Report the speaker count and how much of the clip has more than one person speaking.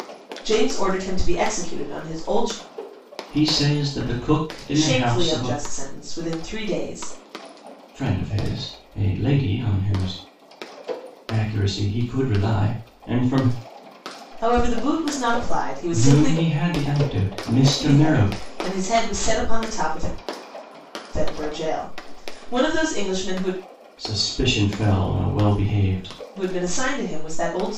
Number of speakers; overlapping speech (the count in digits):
2, about 6%